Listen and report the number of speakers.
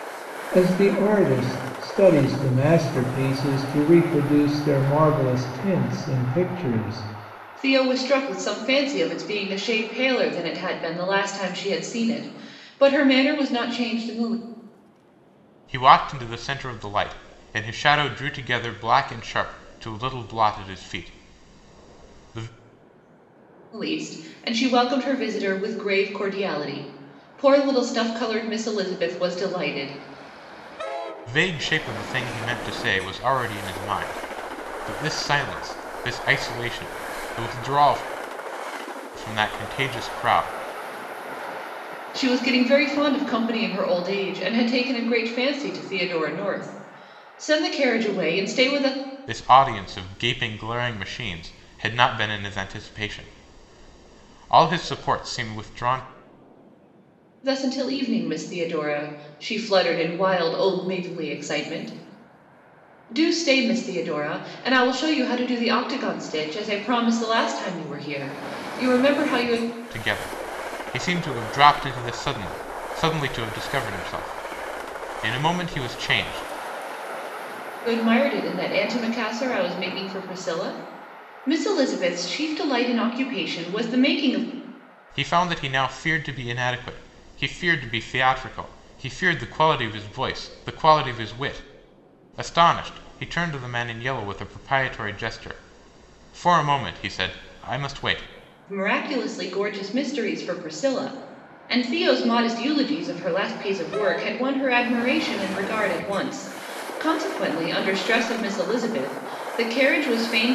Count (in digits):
3